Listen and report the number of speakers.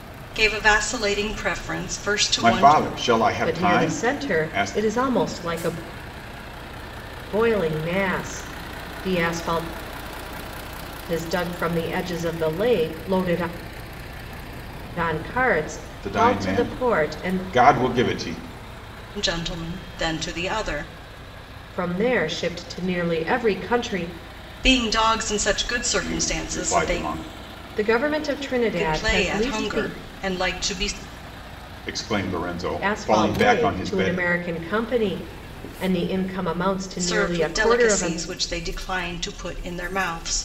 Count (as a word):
three